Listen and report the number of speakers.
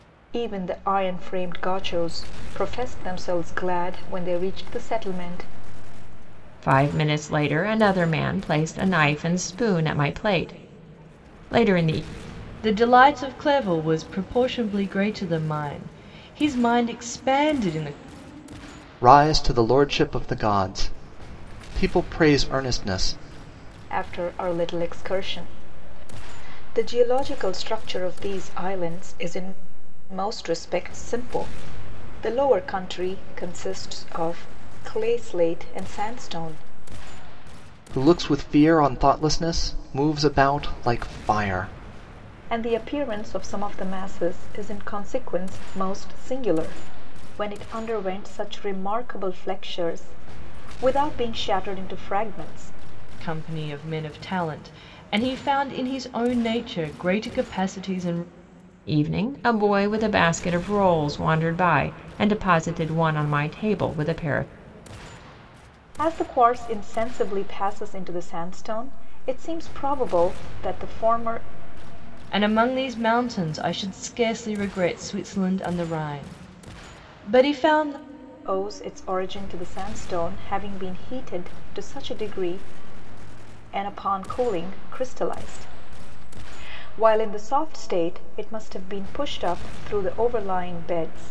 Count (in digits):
4